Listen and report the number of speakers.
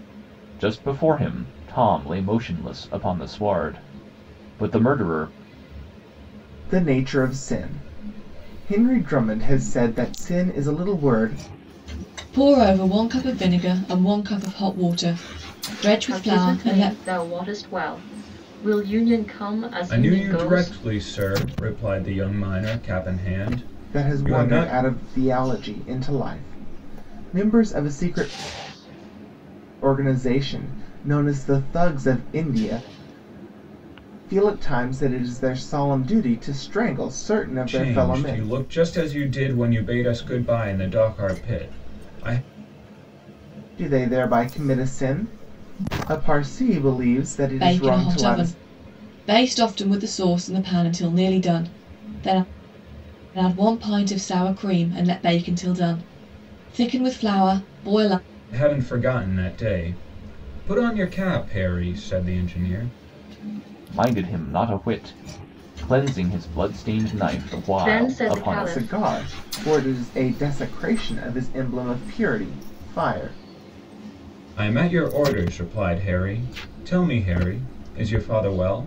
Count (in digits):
5